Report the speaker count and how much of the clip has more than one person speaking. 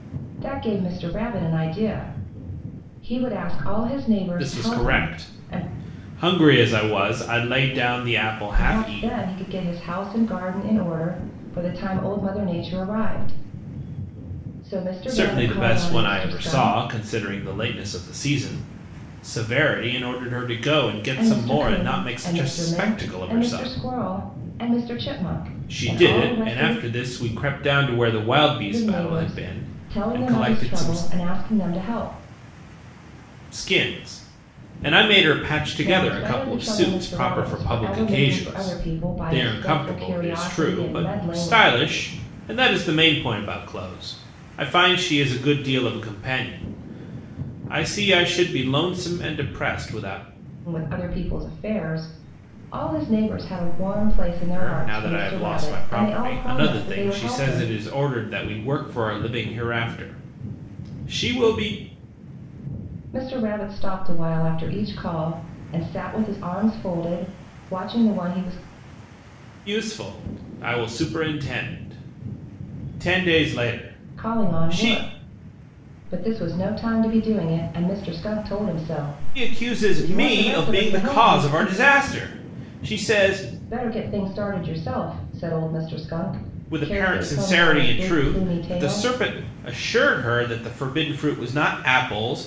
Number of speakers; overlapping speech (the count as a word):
two, about 26%